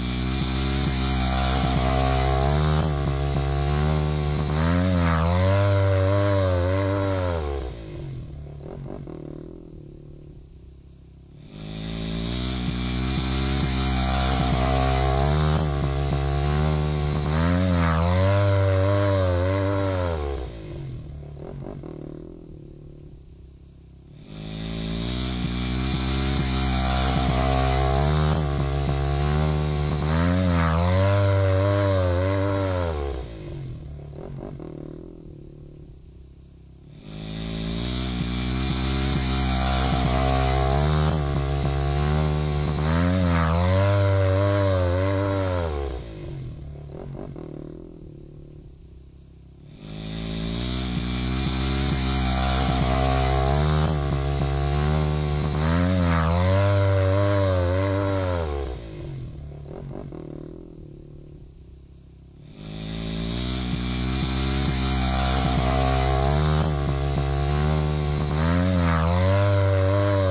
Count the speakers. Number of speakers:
0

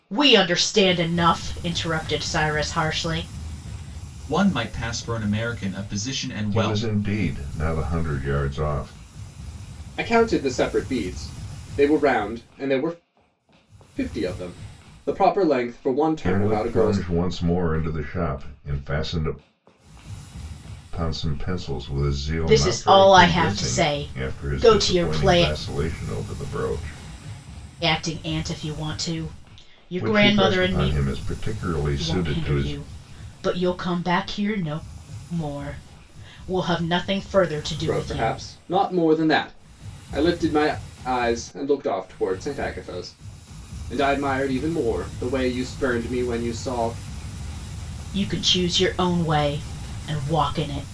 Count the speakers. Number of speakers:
4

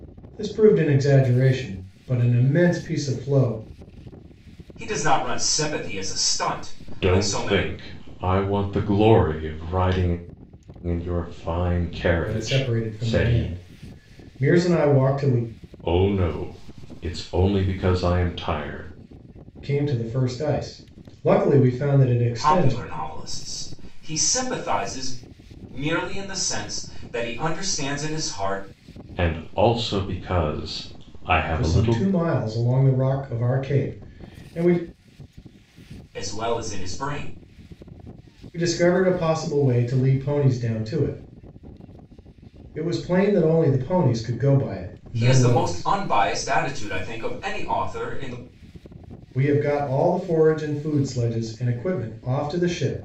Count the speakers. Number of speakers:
3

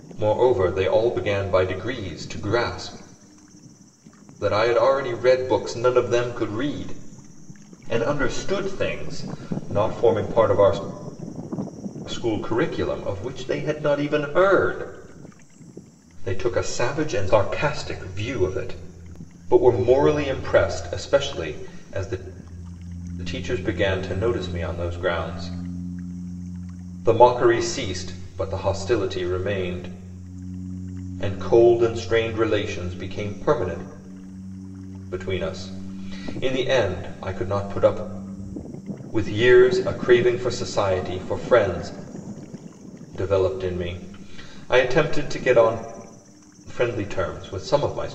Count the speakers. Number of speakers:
1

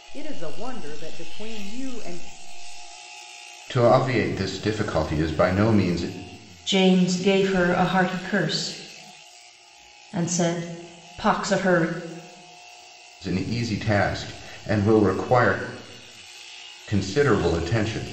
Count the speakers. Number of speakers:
3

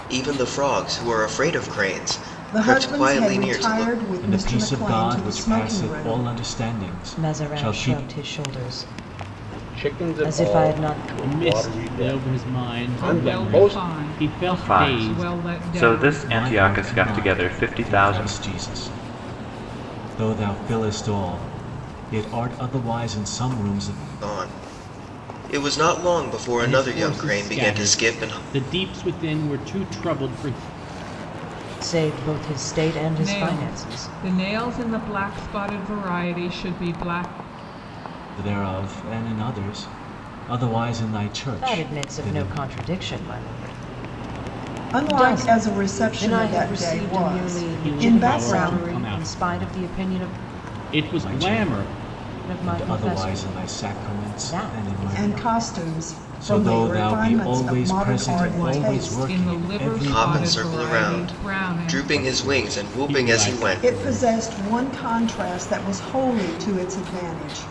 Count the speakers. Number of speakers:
8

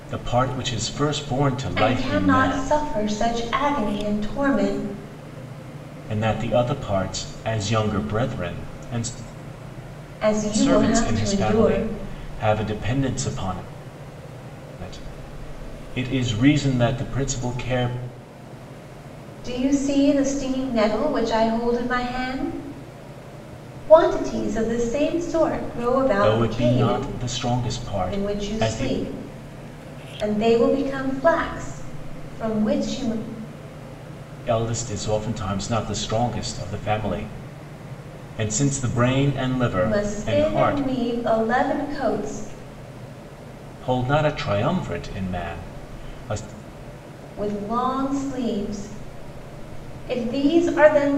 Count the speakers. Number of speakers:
2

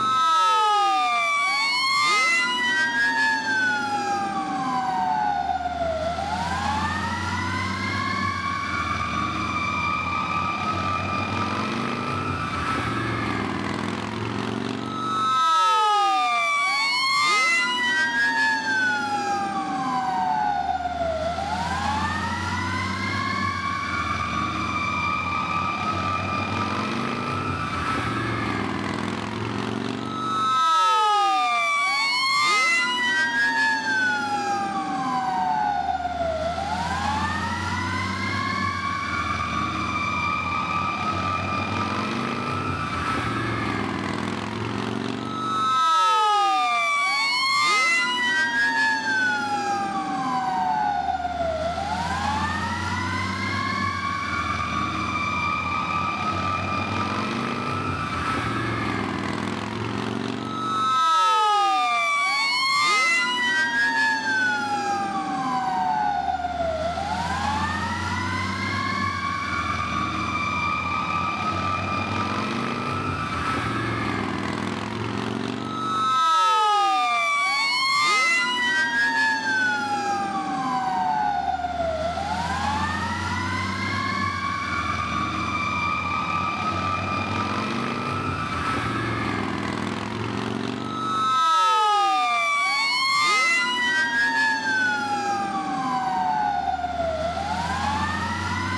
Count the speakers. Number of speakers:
0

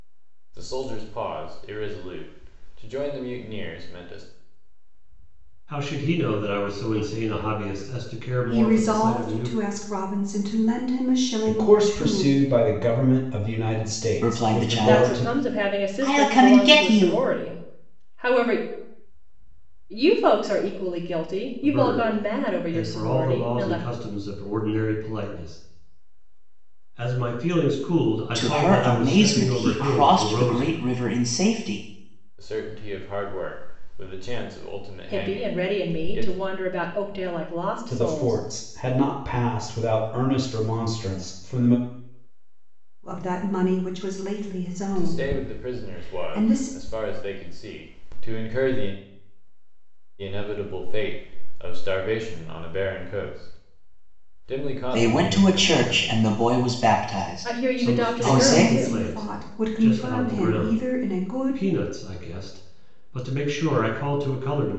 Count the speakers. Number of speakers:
6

